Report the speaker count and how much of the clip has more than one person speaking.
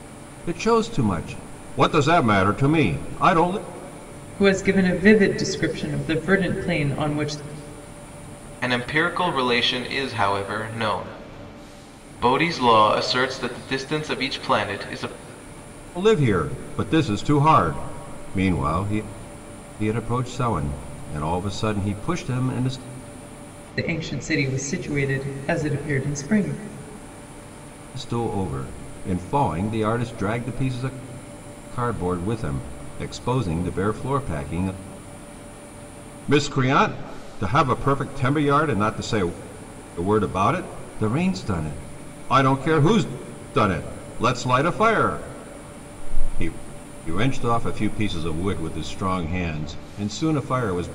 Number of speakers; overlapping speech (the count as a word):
three, no overlap